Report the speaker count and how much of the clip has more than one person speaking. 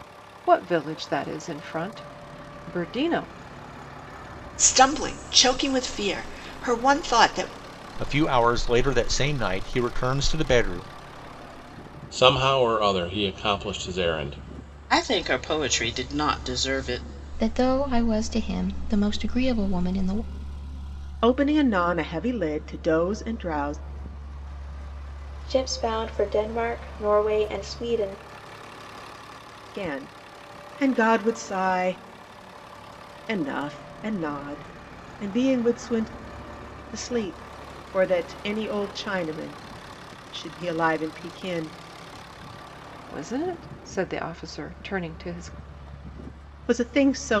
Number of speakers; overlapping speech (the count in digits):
8, no overlap